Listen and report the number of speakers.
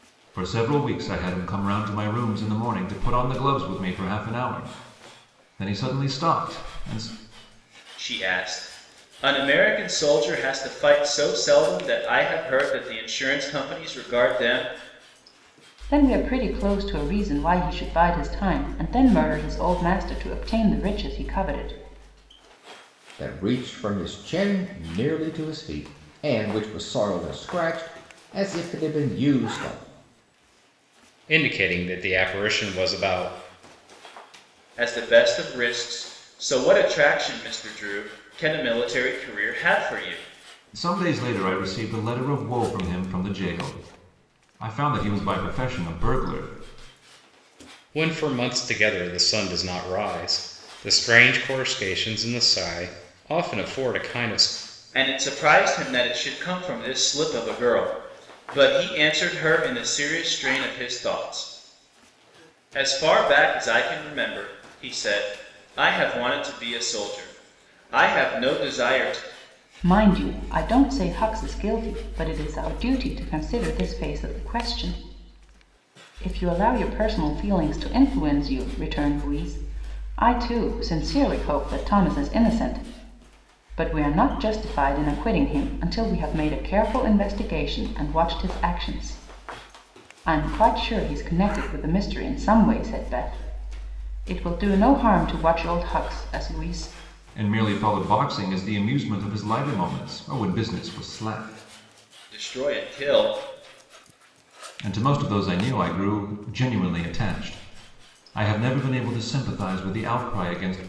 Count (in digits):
5